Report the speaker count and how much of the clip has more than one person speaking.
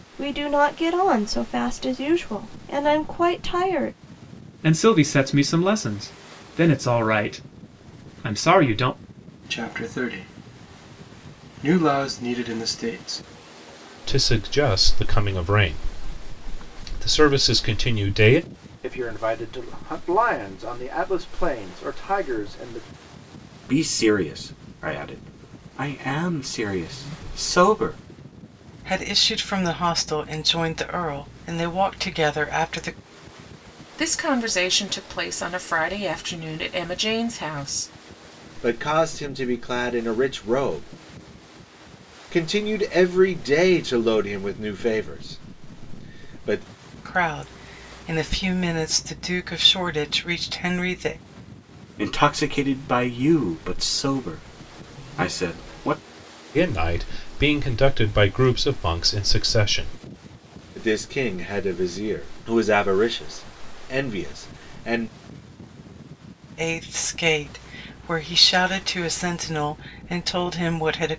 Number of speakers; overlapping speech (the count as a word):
nine, no overlap